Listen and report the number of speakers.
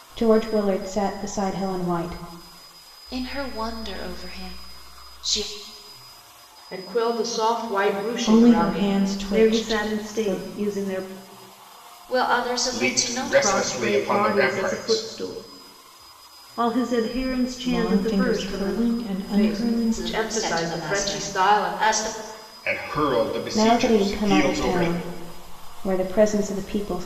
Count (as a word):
seven